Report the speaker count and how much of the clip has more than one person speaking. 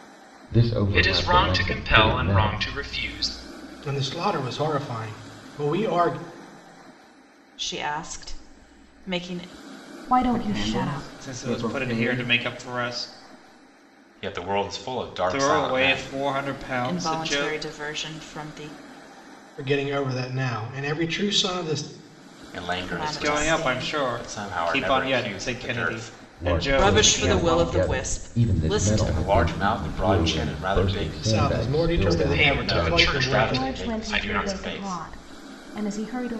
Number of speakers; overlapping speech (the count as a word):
eight, about 47%